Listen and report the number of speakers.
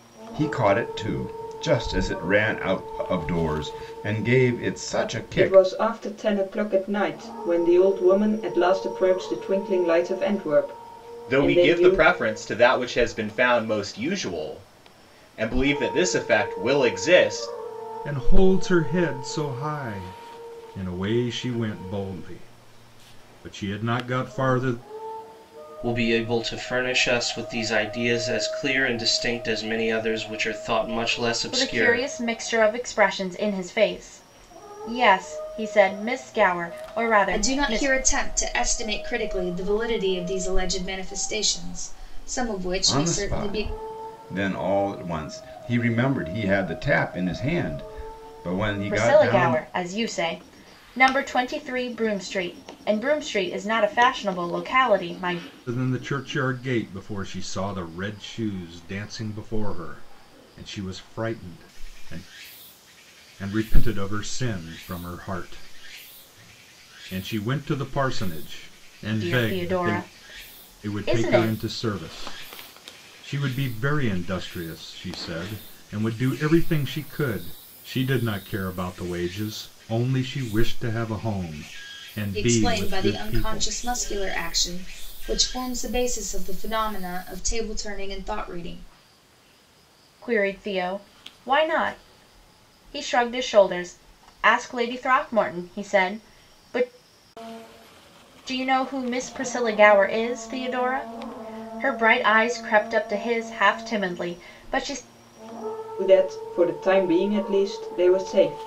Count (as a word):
seven